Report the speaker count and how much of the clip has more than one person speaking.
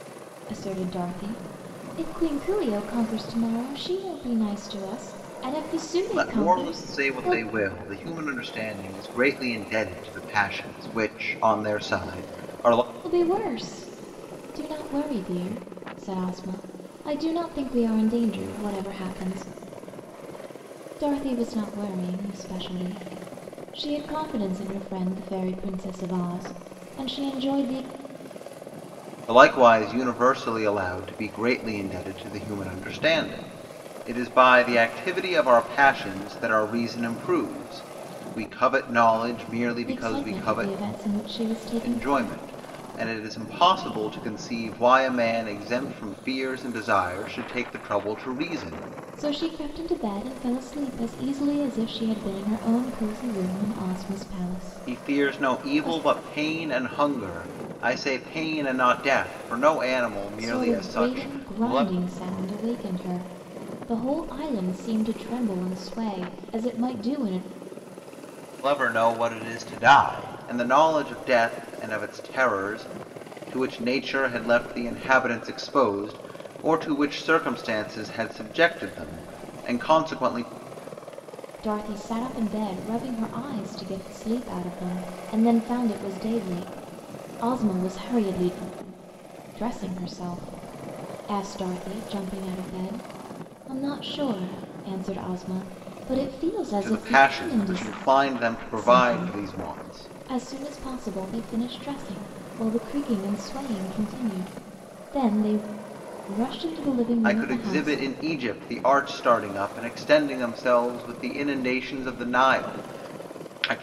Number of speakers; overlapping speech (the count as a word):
two, about 8%